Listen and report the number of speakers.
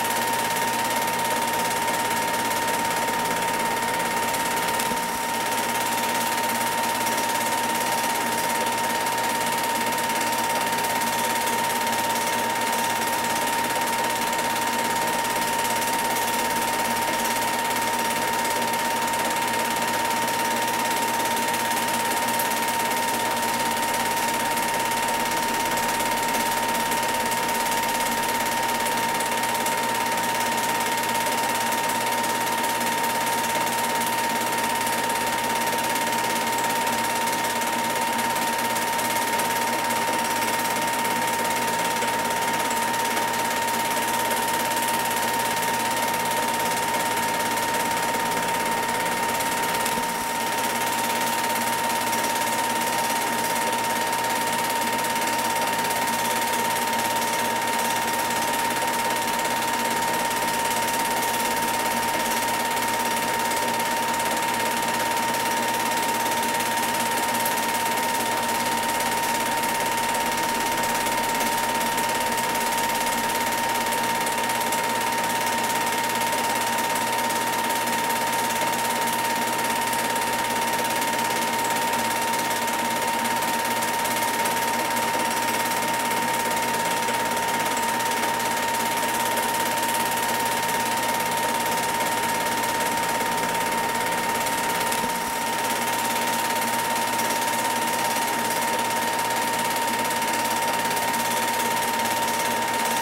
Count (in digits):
0